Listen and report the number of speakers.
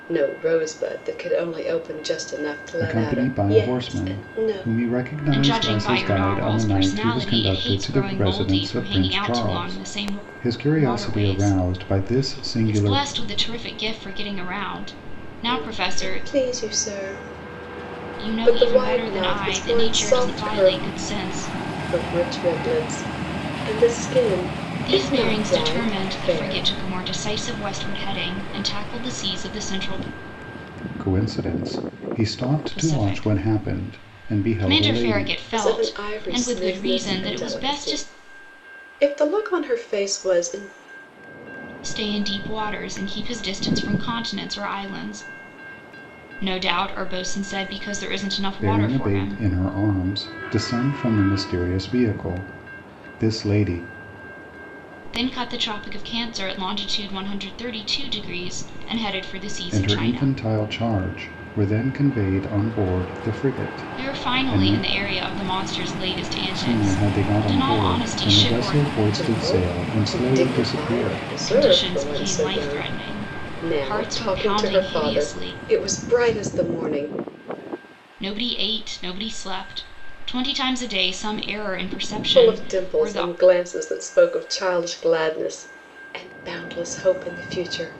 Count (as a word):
three